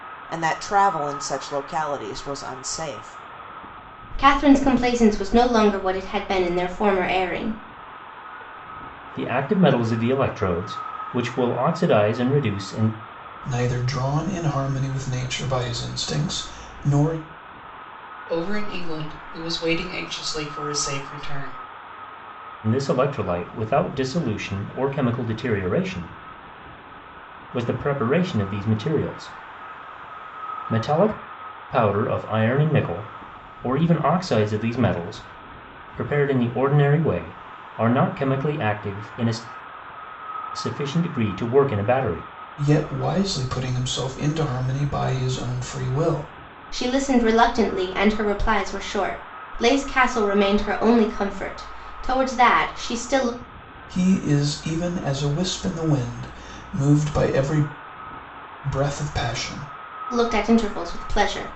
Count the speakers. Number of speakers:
5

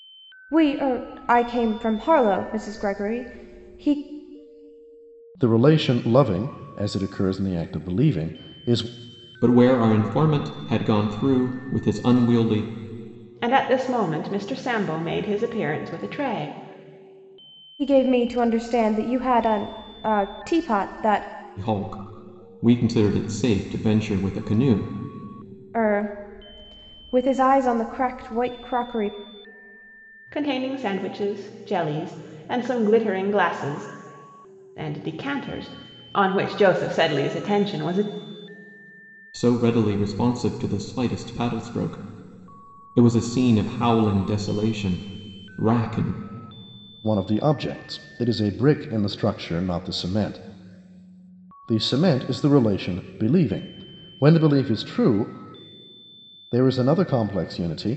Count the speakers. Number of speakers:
4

